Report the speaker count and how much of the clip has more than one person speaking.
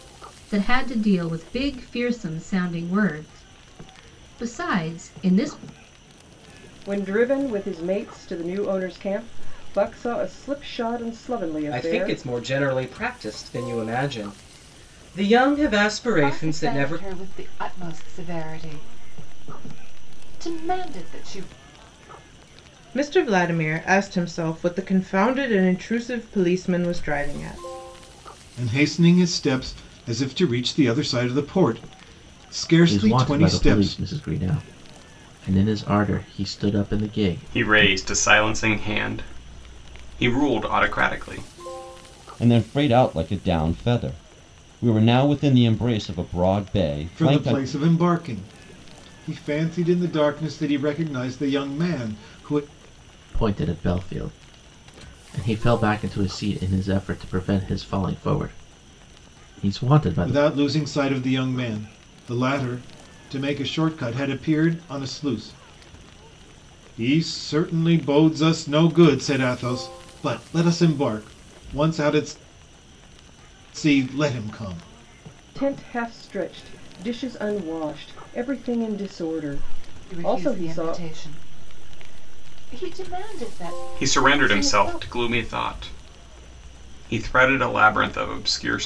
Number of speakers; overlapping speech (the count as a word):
nine, about 7%